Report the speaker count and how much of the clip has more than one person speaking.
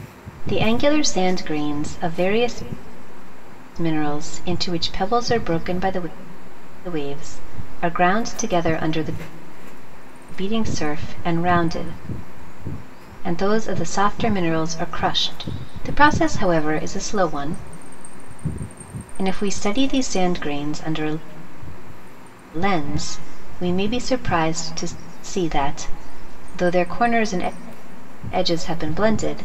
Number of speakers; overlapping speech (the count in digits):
1, no overlap